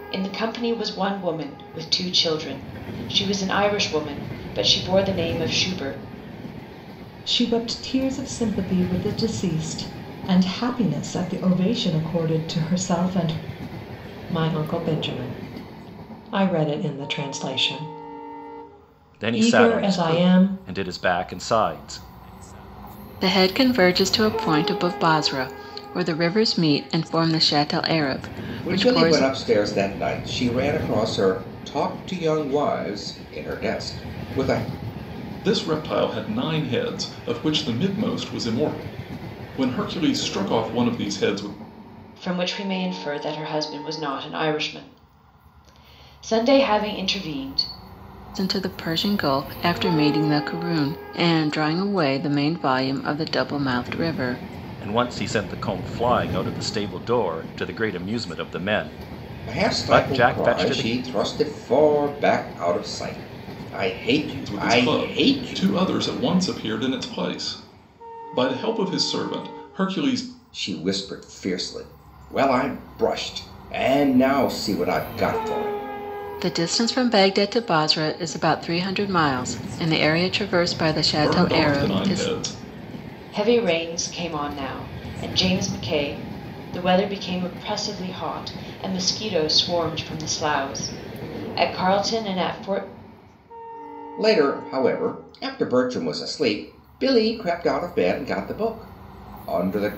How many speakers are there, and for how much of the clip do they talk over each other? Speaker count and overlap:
seven, about 6%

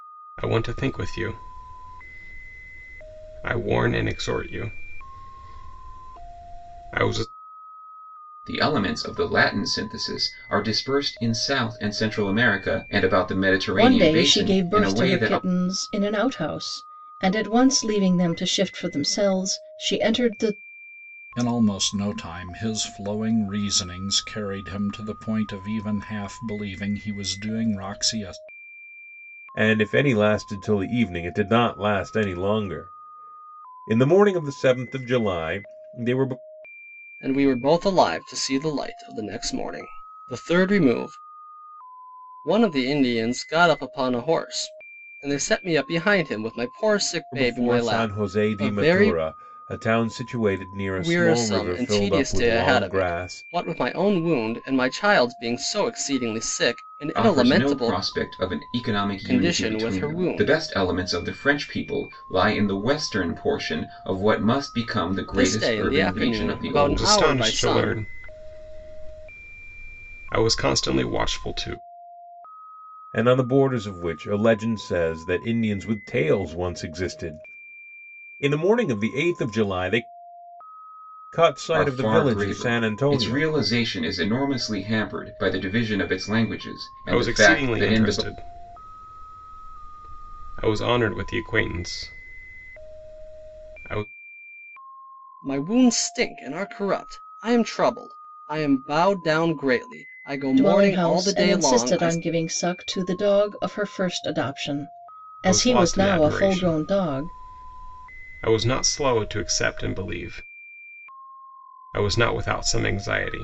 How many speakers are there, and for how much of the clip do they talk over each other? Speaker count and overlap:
six, about 15%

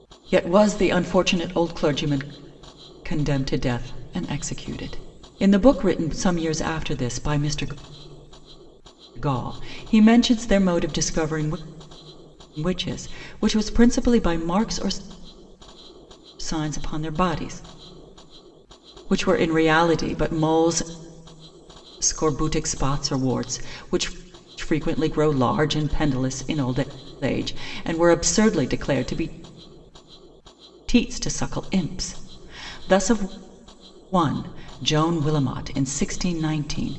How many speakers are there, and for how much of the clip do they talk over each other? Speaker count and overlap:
one, no overlap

